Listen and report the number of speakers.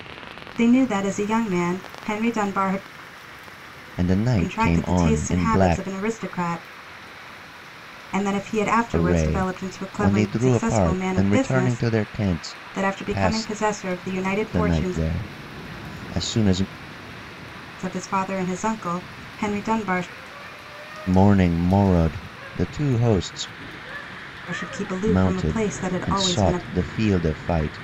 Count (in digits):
2